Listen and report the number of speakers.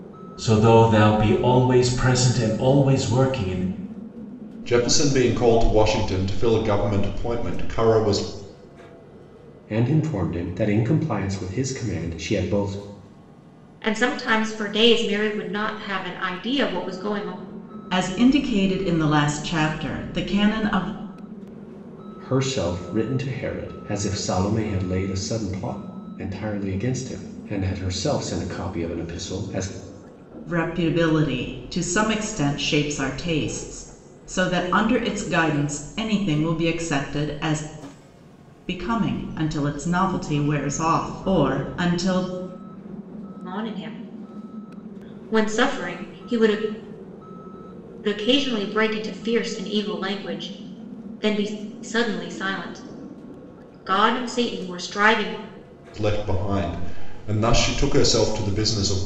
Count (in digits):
5